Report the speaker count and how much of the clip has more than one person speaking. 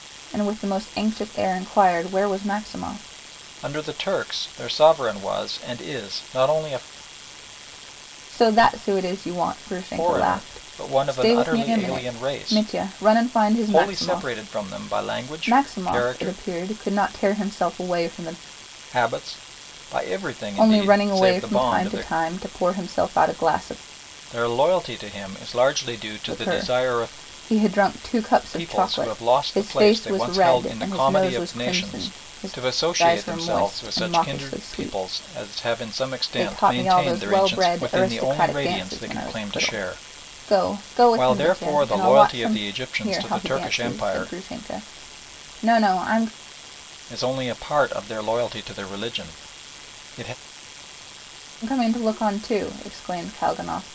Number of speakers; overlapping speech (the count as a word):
two, about 37%